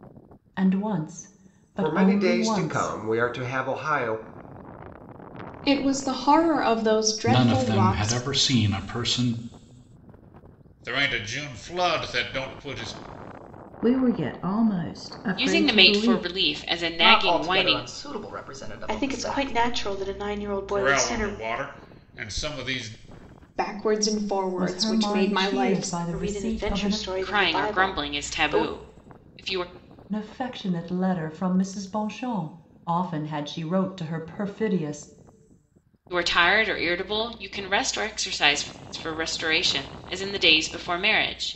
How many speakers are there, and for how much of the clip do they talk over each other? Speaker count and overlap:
nine, about 22%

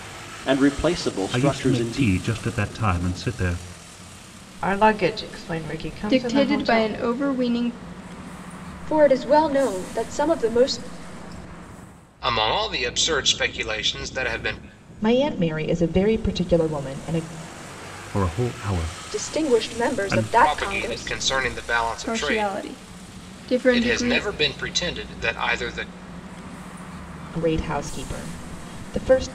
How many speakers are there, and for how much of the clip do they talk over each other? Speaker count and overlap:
seven, about 18%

